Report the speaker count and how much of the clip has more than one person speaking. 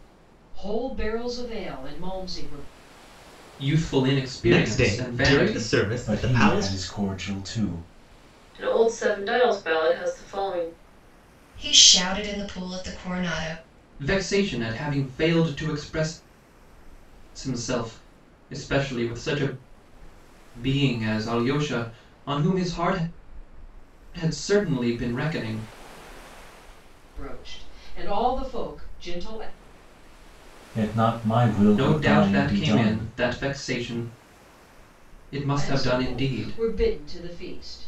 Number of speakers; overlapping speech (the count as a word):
six, about 12%